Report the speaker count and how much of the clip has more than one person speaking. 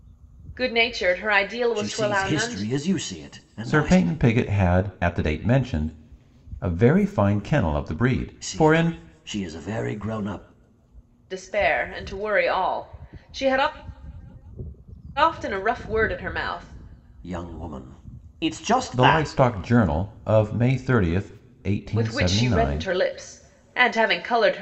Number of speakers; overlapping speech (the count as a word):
three, about 14%